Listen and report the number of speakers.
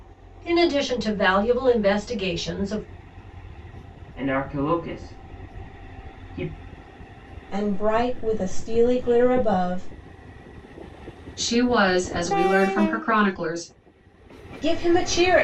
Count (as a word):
four